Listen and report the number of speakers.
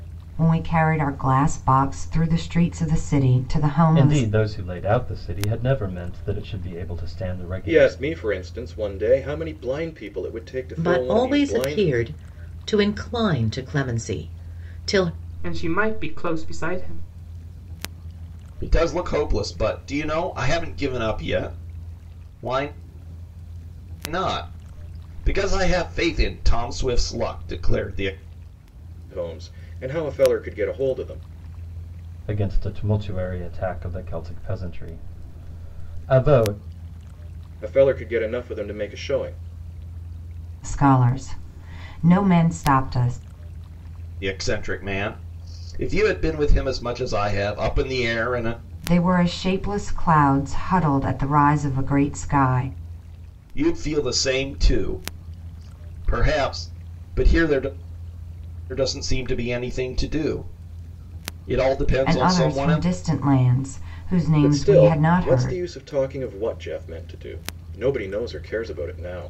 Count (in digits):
6